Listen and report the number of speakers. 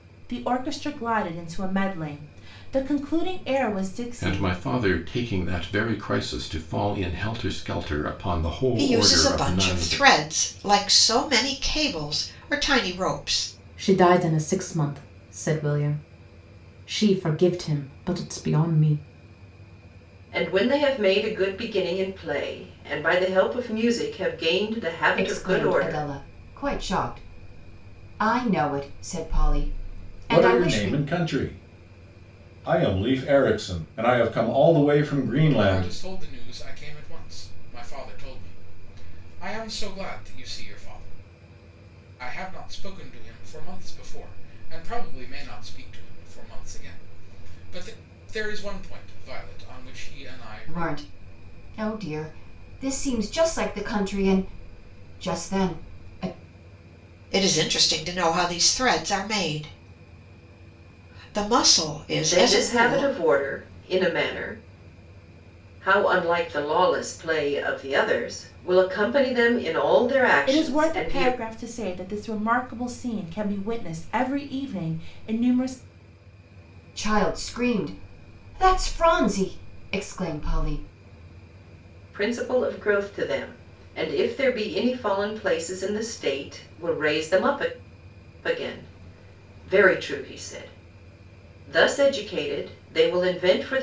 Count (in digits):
8